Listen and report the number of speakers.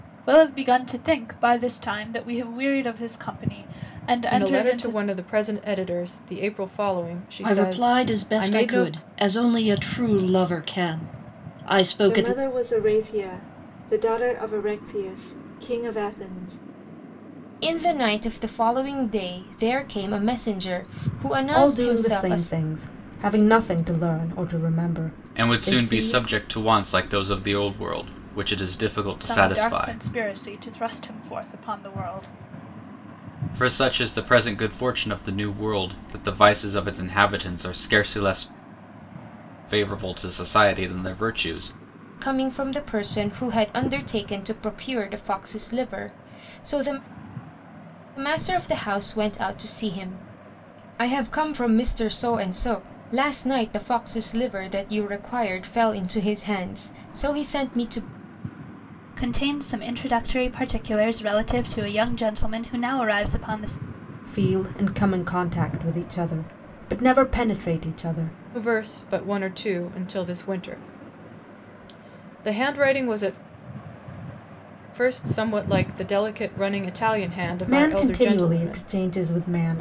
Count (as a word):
seven